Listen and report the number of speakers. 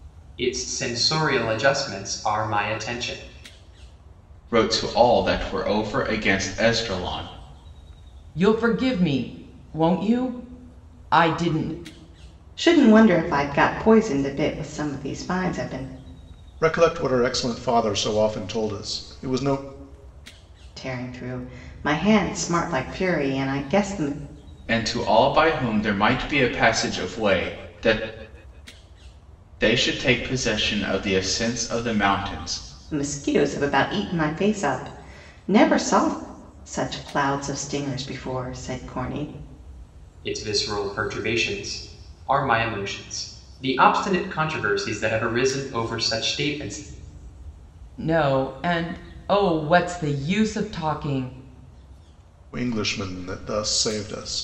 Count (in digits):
5